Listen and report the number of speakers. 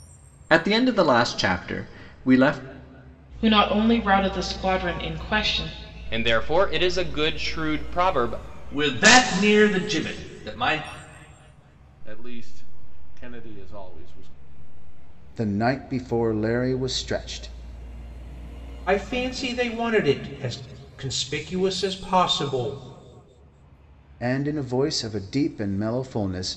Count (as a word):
seven